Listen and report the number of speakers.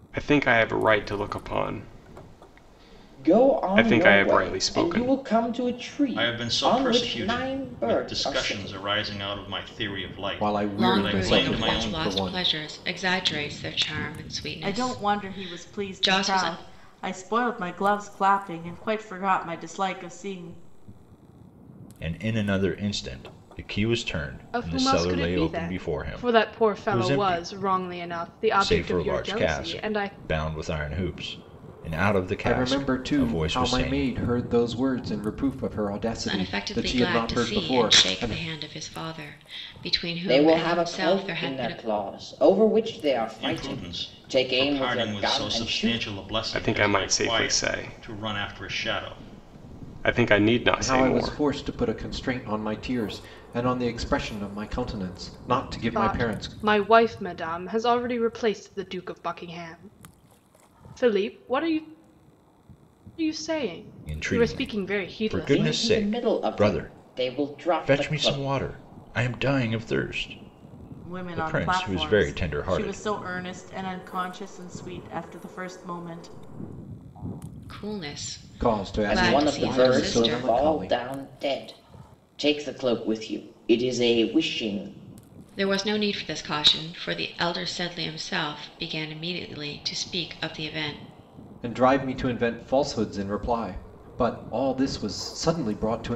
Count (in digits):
8